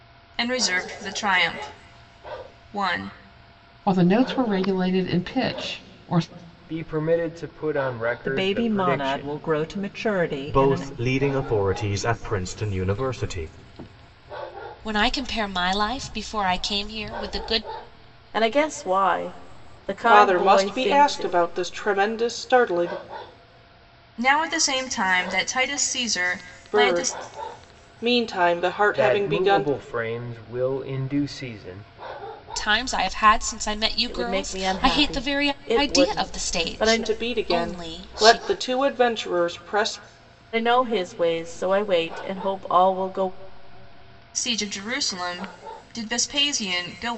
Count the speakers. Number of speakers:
8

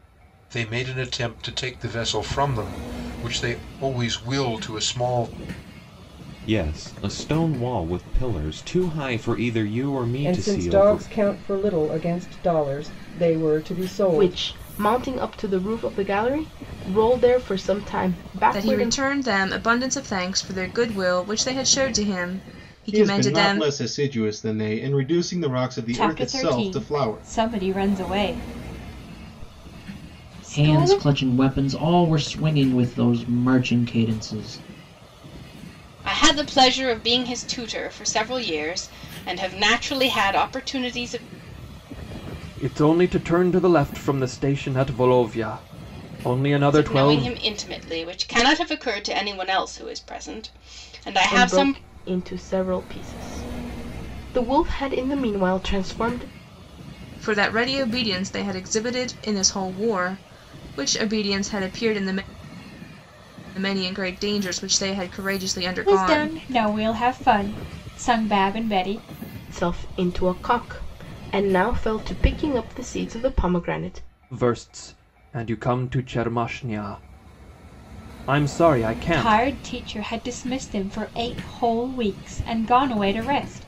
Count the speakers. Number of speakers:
10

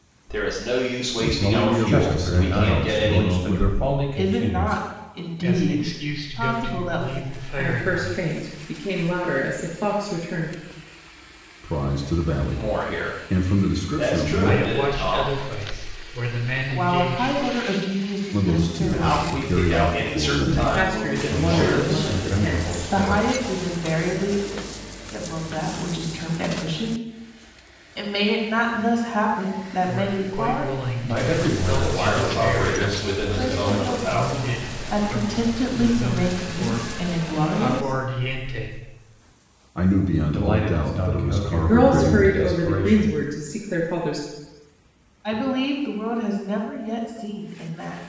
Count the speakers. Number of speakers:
6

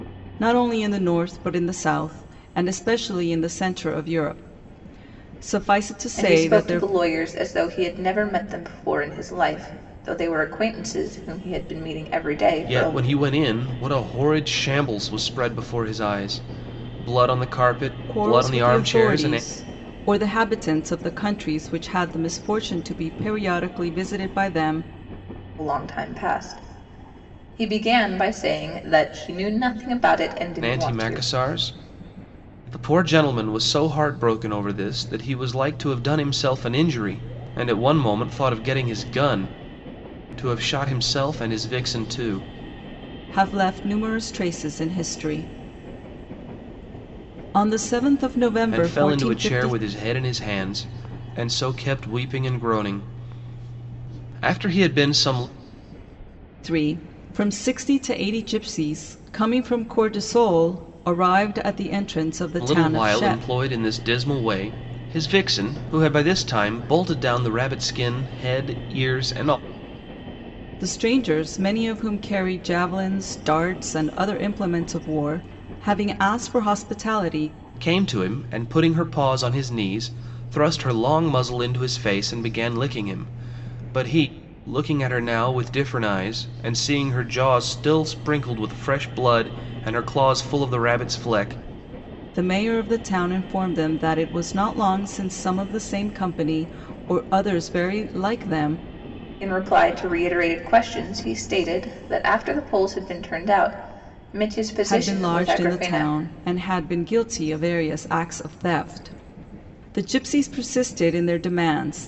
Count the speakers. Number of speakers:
3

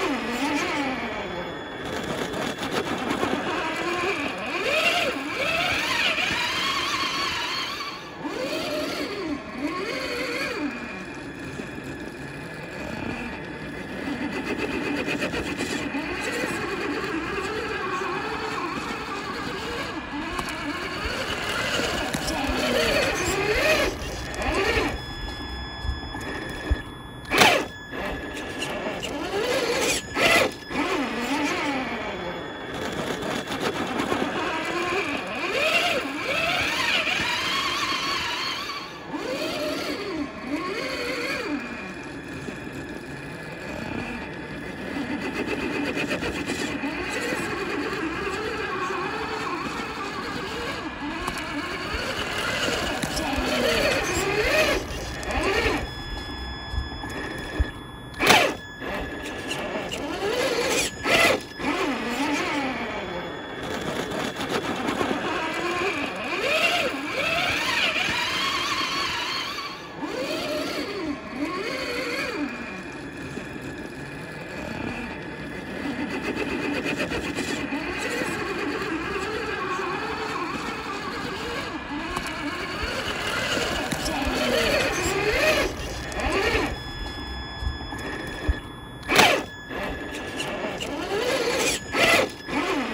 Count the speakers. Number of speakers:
0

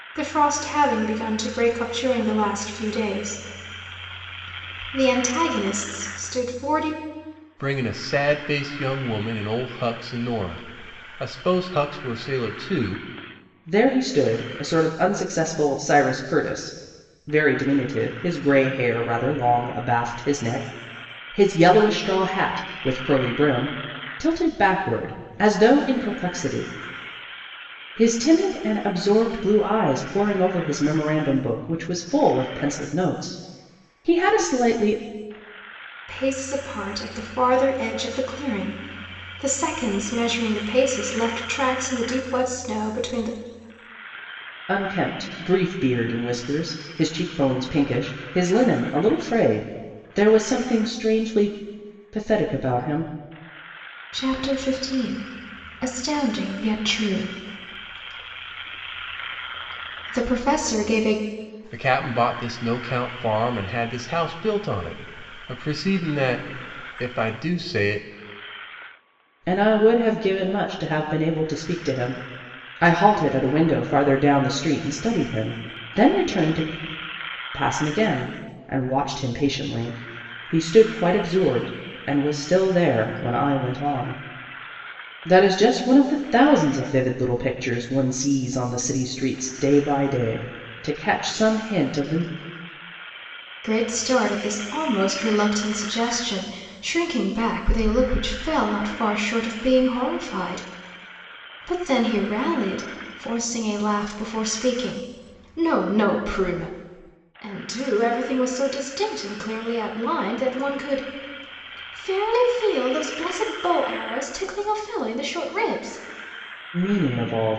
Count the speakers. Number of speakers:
3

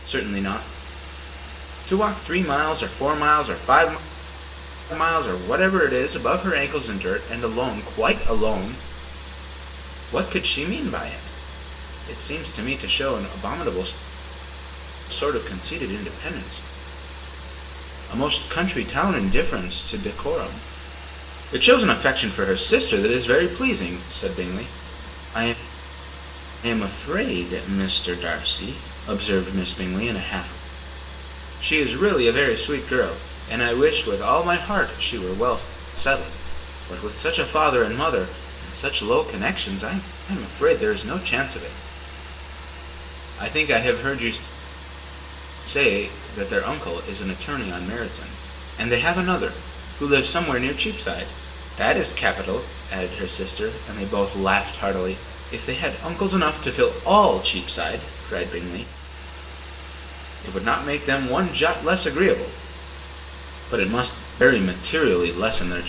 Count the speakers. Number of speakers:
1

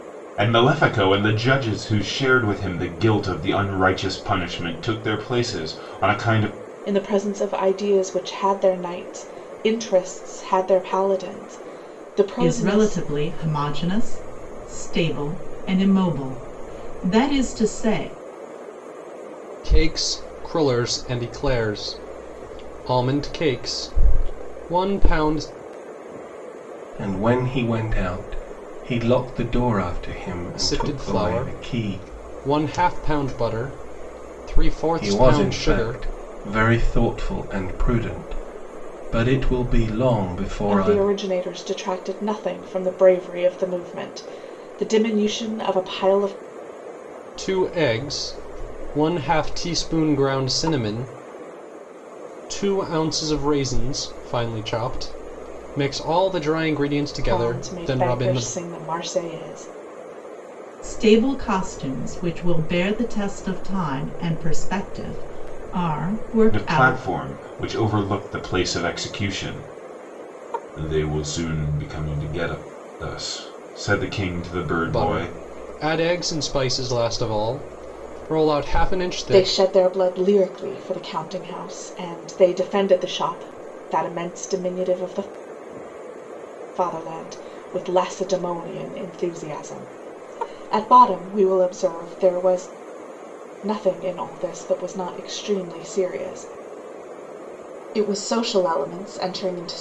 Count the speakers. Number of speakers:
5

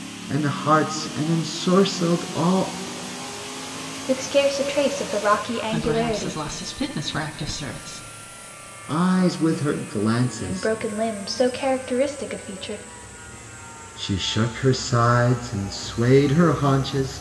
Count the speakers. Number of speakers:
3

